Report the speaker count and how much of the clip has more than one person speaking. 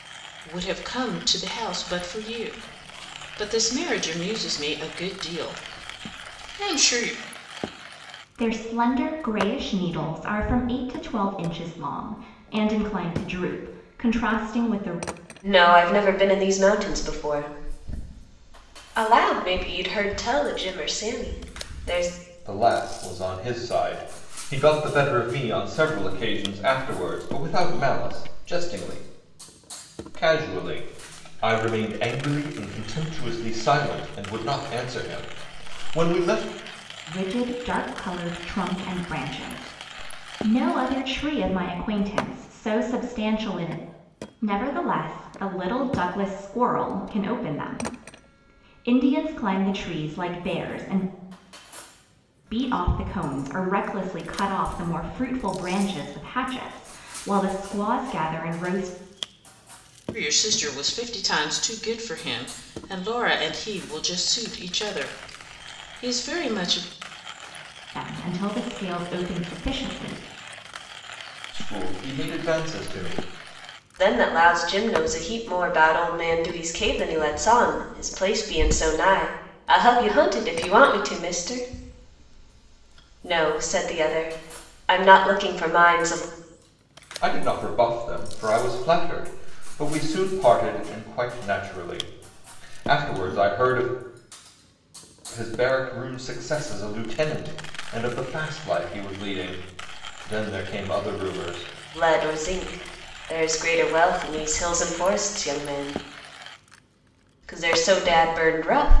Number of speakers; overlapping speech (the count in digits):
4, no overlap